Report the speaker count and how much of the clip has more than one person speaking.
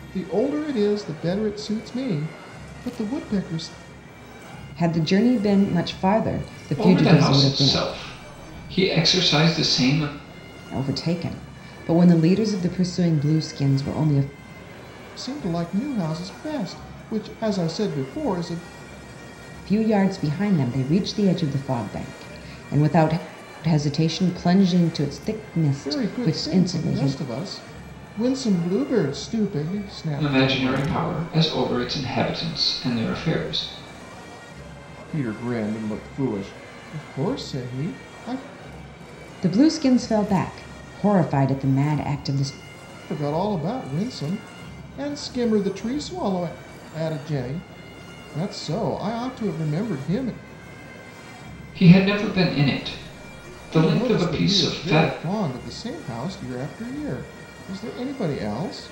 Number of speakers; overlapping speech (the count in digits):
3, about 8%